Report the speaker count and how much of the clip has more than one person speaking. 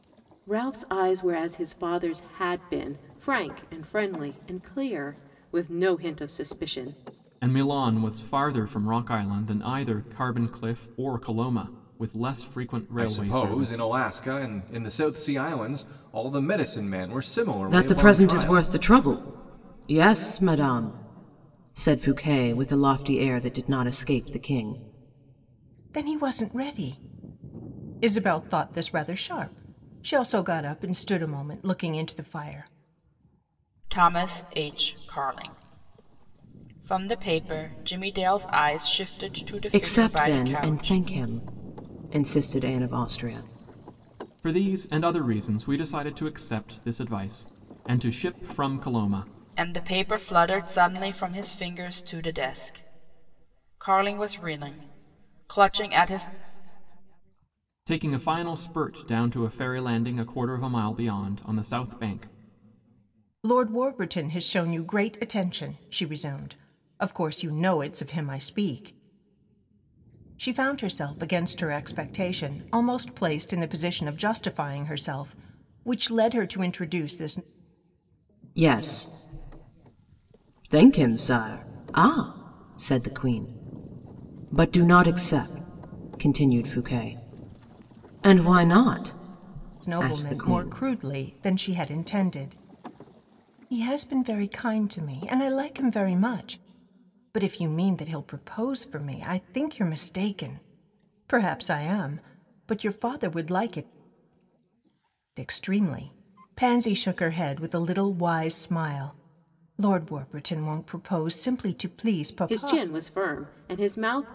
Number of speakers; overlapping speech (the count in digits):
6, about 4%